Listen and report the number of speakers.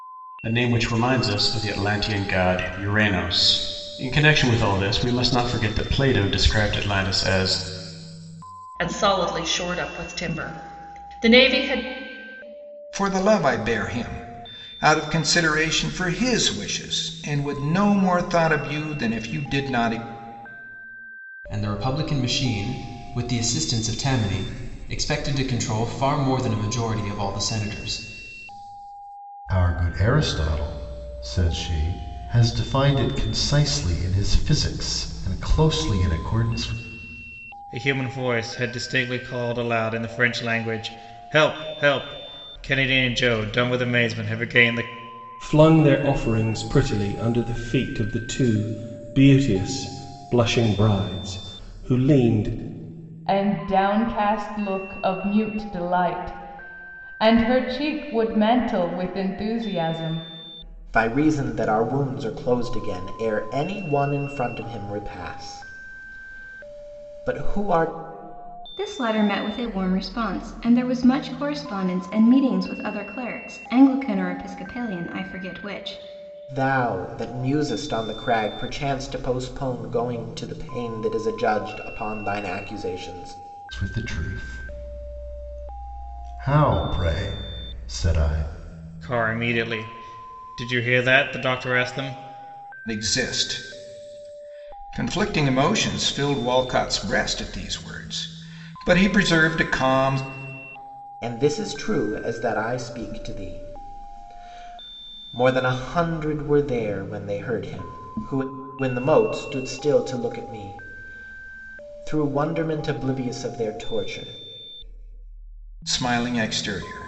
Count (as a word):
ten